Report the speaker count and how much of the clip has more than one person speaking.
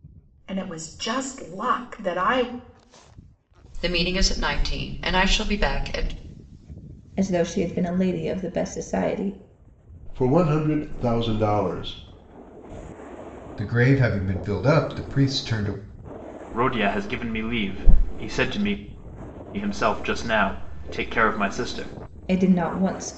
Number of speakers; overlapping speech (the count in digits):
6, no overlap